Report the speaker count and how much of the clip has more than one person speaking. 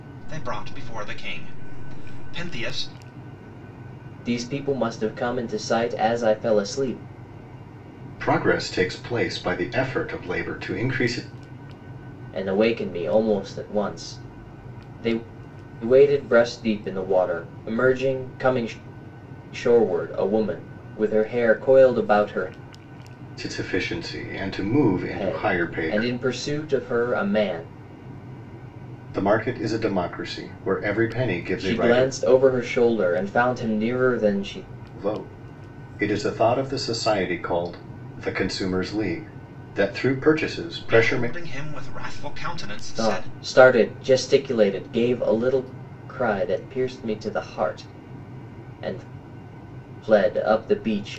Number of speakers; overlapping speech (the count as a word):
three, about 5%